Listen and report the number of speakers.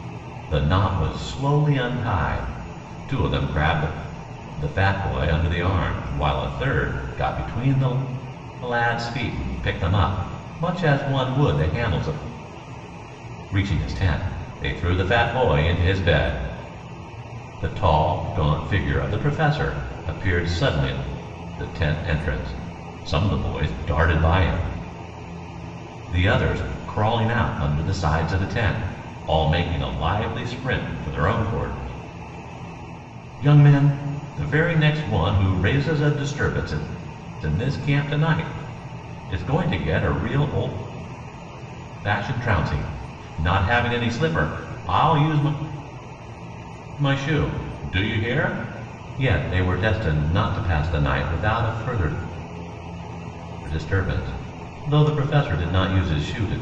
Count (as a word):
one